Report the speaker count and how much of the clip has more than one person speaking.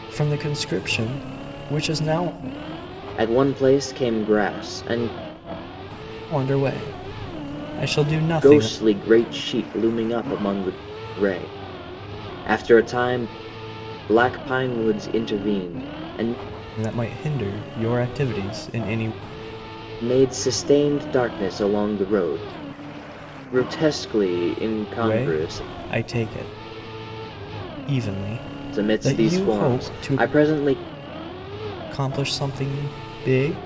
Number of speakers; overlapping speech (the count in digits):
2, about 7%